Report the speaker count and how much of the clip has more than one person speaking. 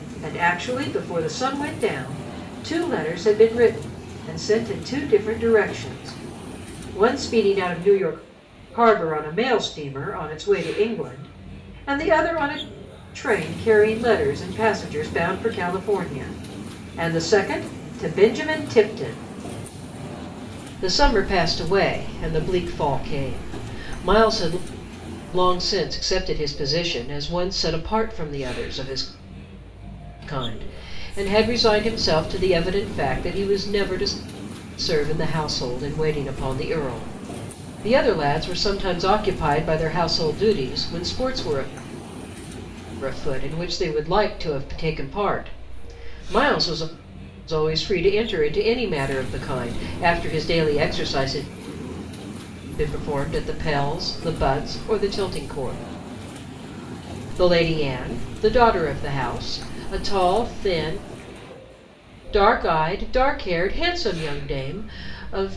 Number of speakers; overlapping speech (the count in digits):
1, no overlap